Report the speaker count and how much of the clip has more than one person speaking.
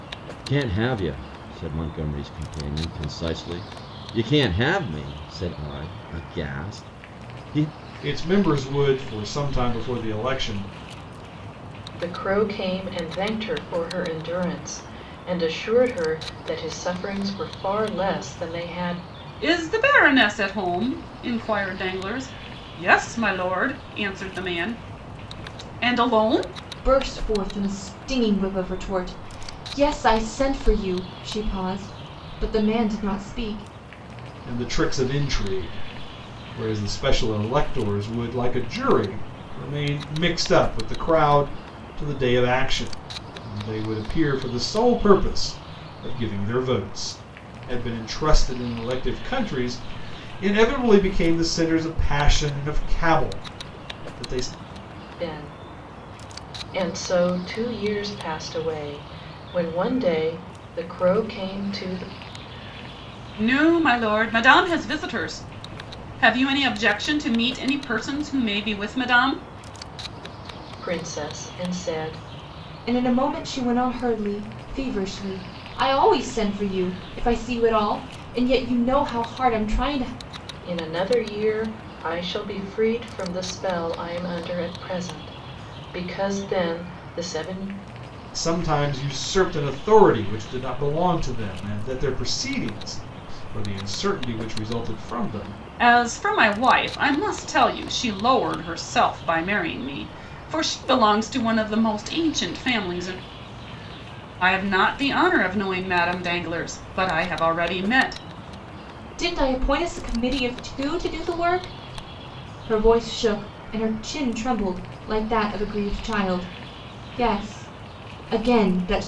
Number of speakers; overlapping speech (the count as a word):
five, no overlap